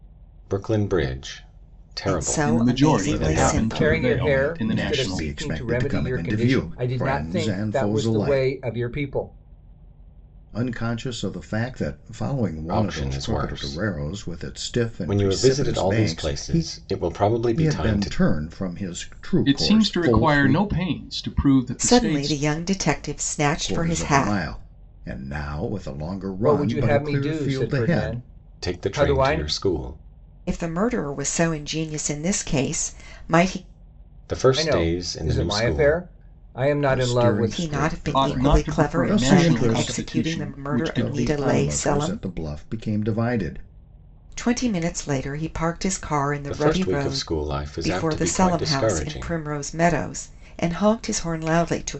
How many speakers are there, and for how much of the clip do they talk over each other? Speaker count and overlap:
five, about 48%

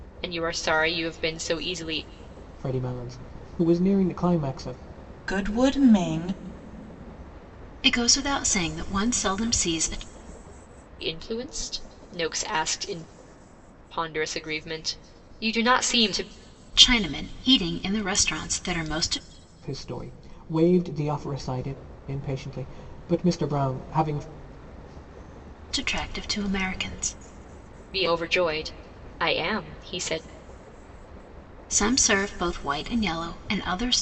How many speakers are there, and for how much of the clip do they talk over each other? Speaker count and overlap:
four, no overlap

